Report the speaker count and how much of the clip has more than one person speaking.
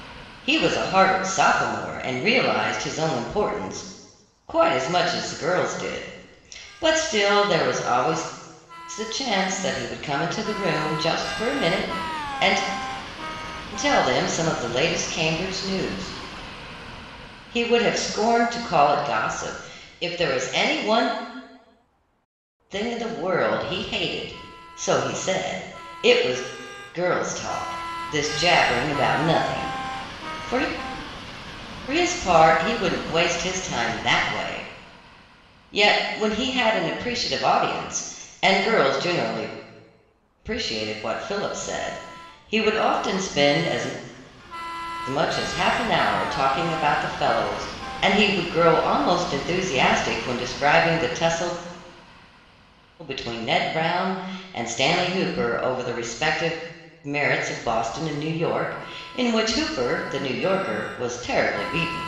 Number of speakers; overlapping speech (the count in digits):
1, no overlap